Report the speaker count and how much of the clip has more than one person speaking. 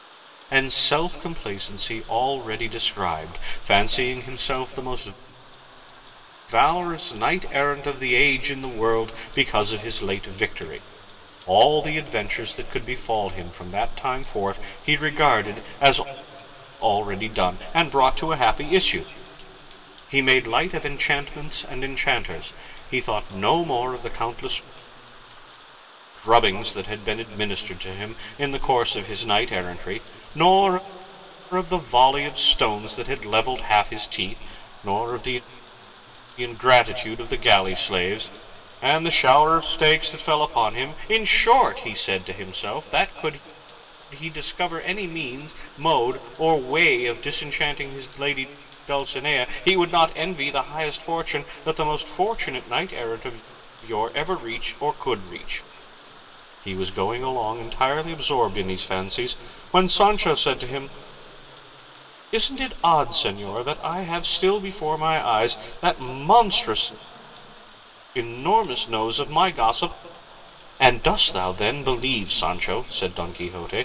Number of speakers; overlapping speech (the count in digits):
1, no overlap